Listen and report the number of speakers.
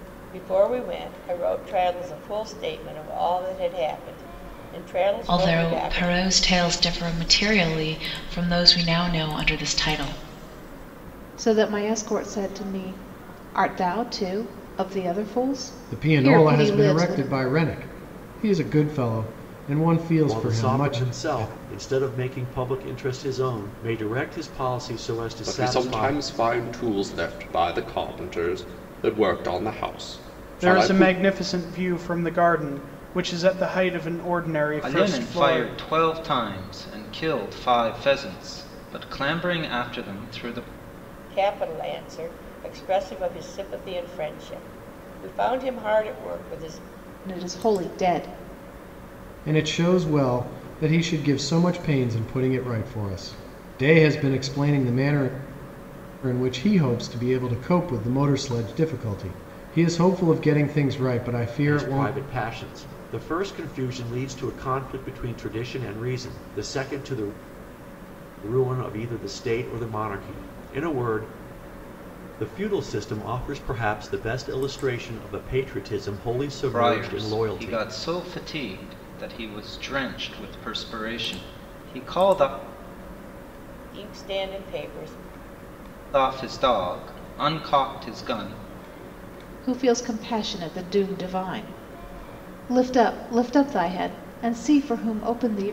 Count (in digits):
8